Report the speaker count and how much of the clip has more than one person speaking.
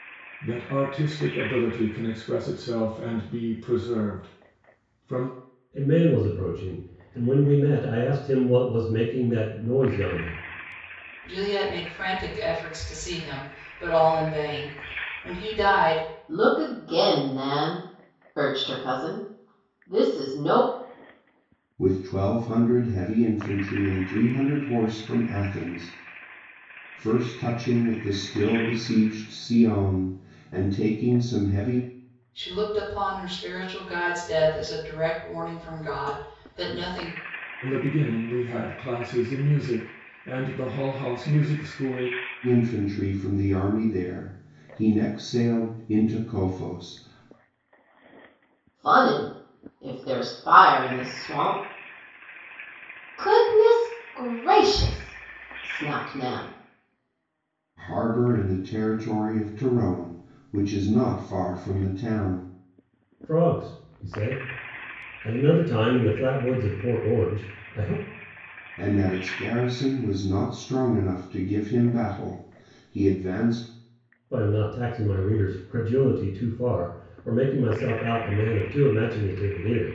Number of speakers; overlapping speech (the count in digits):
5, no overlap